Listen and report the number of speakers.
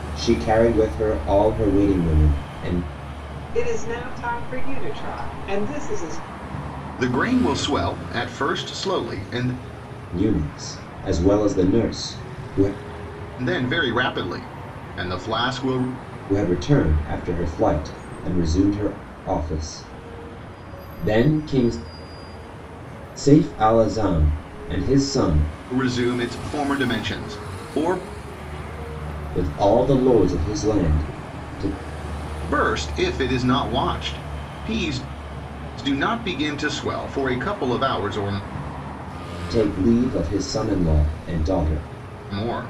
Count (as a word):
three